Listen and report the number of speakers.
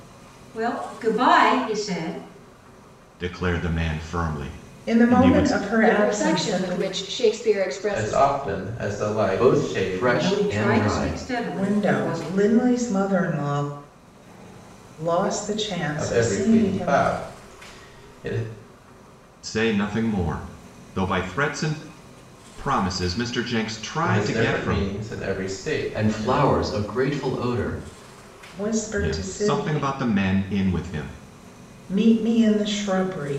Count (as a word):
six